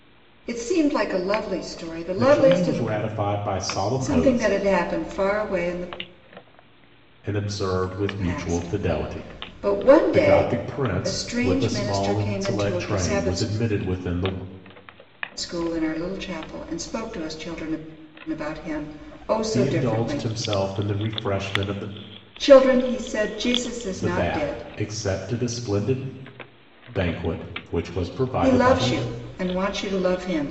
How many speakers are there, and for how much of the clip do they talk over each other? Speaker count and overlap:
2, about 25%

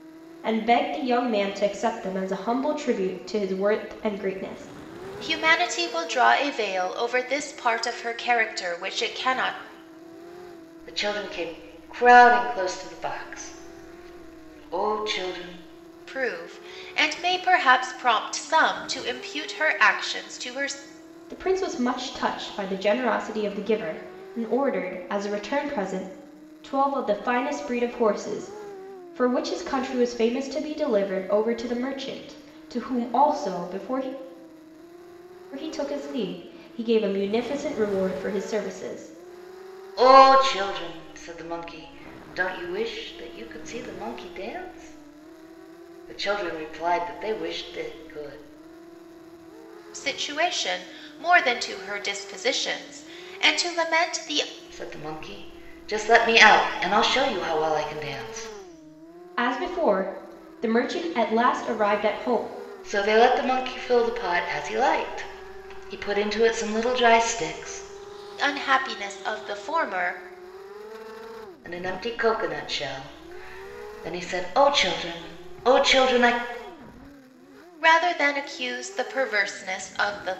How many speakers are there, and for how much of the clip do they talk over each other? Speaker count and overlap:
3, no overlap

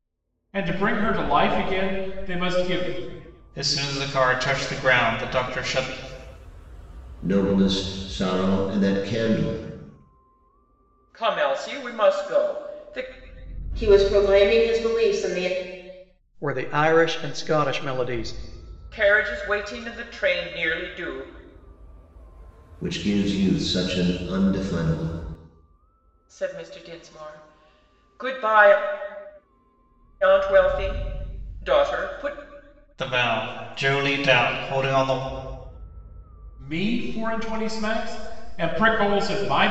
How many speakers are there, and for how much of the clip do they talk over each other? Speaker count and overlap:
6, no overlap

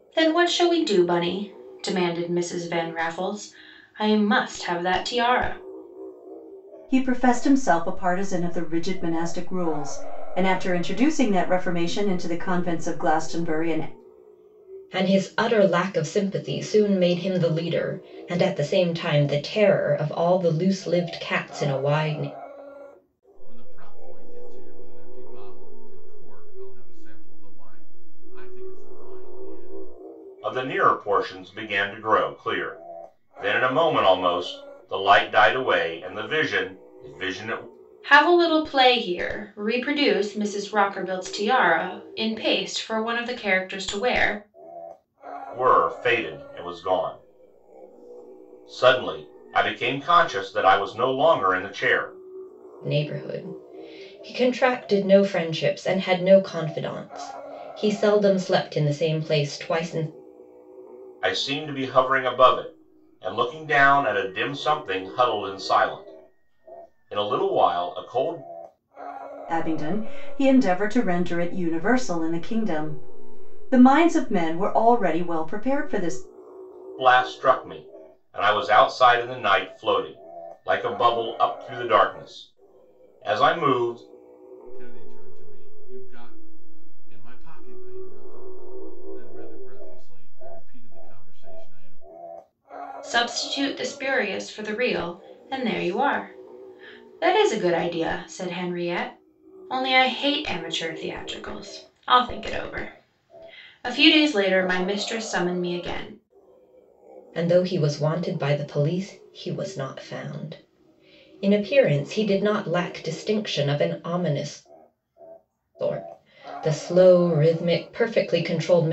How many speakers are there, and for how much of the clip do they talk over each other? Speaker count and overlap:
5, no overlap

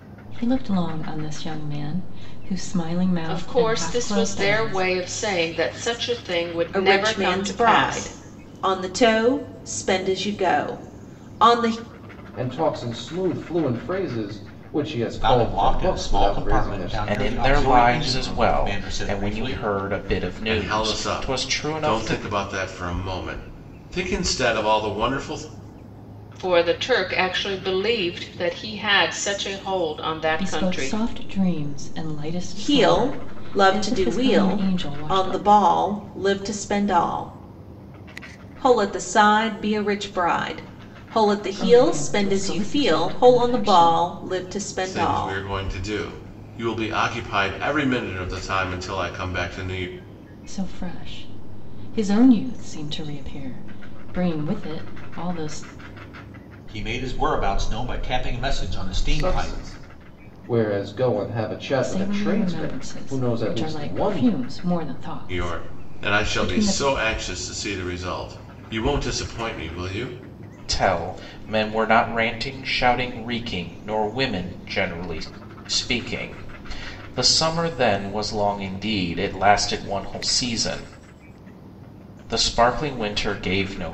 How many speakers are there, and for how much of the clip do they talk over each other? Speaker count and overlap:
7, about 24%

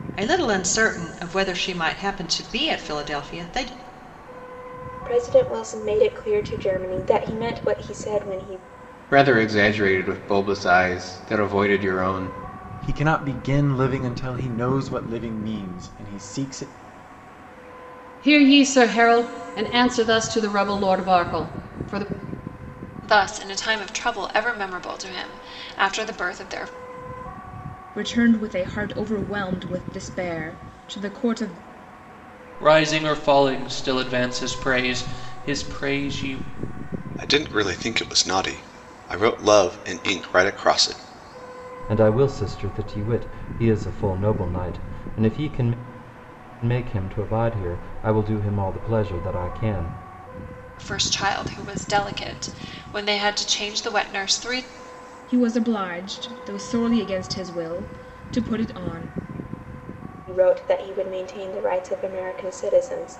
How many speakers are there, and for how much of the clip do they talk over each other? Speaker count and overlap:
10, no overlap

